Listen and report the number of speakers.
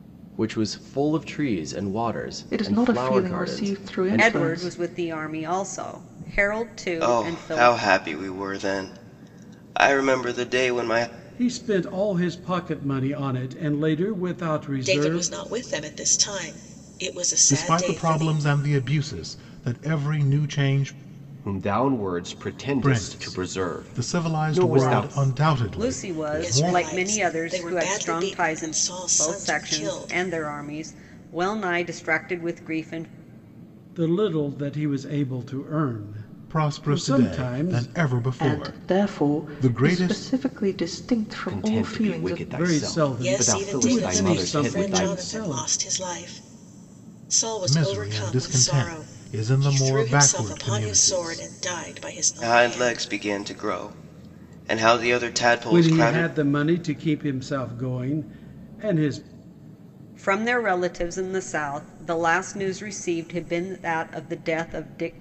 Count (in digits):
8